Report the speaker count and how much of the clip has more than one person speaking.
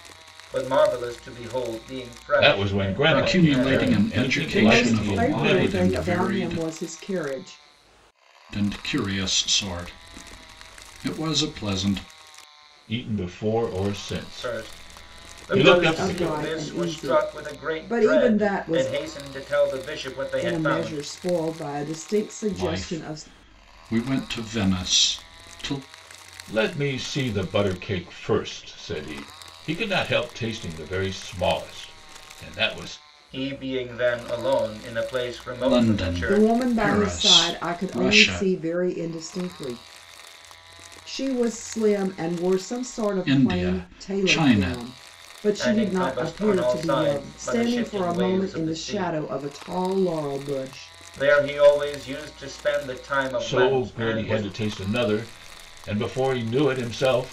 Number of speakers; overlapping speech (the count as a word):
four, about 34%